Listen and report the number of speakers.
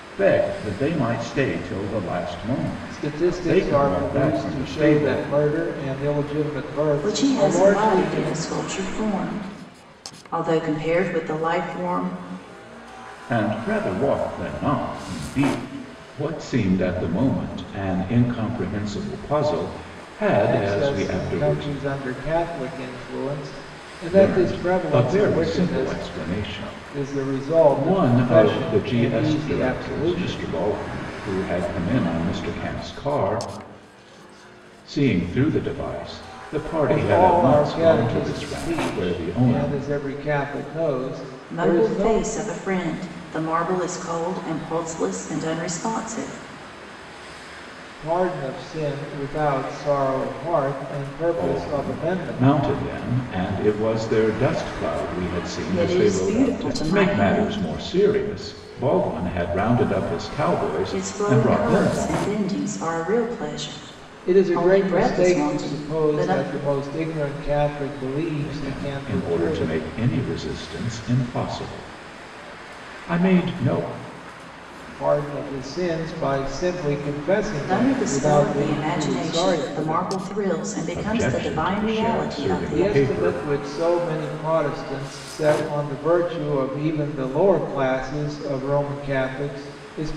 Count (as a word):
three